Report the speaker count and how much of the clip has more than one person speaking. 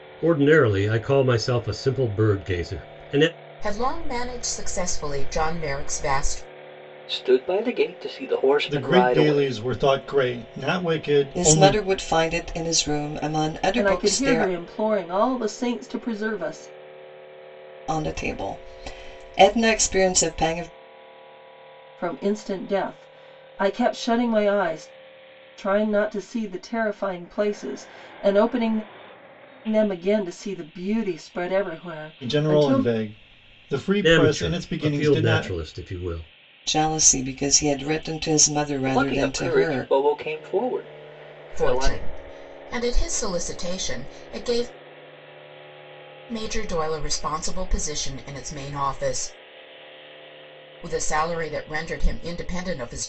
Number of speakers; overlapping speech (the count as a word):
six, about 11%